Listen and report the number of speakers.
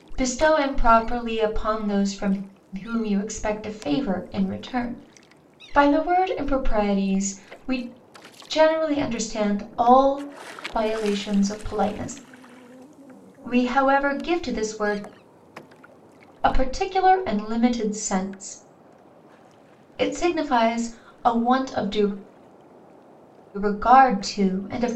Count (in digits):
1